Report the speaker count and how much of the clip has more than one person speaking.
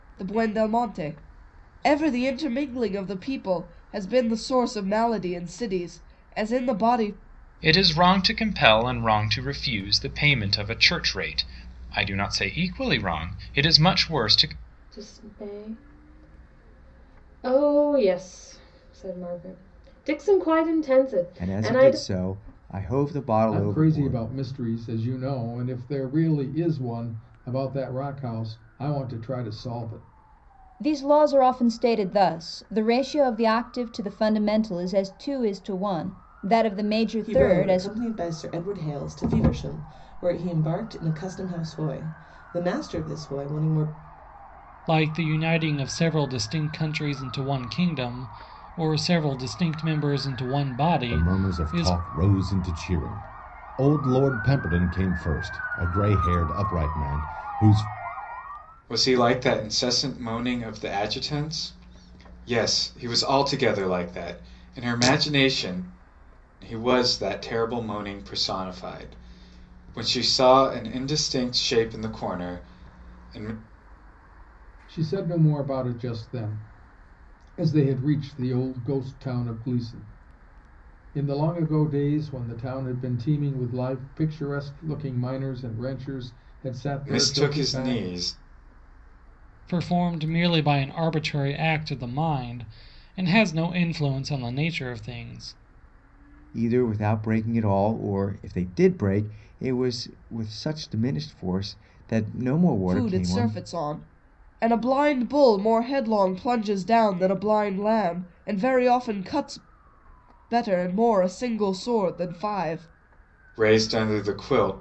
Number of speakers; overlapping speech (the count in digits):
10, about 4%